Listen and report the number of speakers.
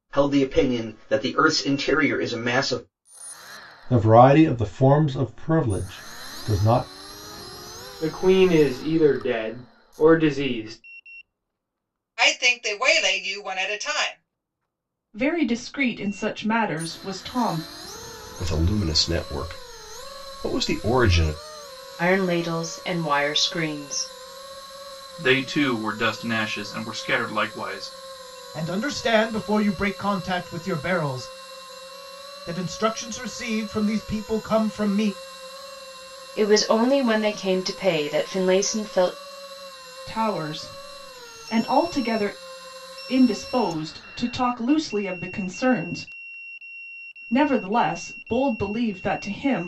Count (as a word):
nine